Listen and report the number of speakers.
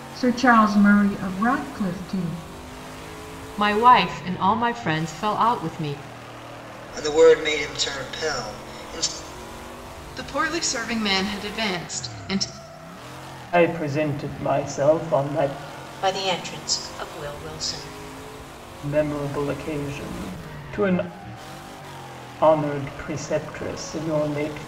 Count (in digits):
6